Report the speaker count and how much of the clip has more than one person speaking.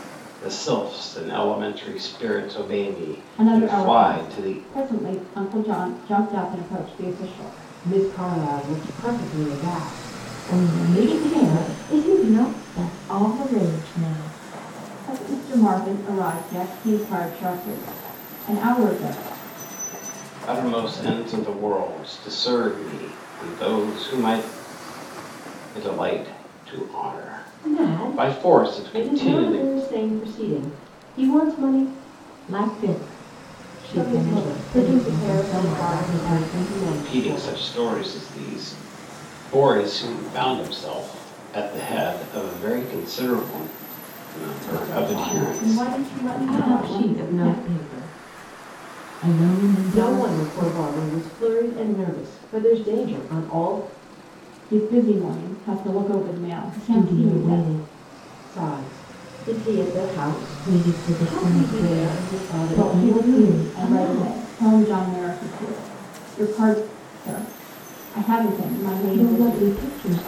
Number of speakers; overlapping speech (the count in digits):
4, about 25%